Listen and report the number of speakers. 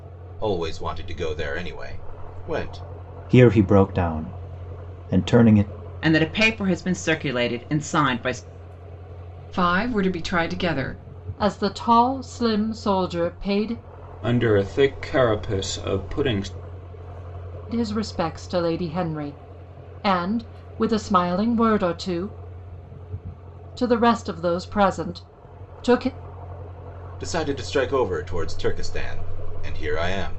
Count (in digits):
6